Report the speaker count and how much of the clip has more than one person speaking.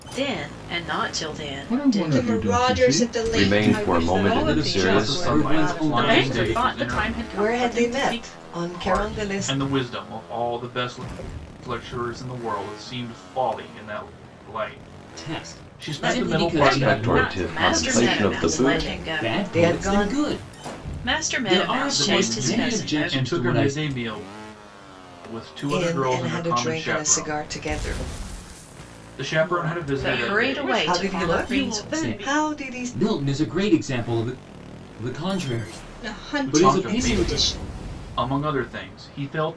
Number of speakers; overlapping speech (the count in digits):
9, about 55%